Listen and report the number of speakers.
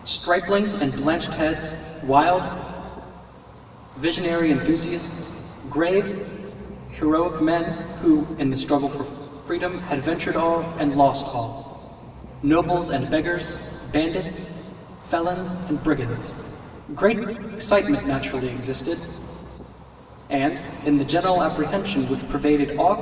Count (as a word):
one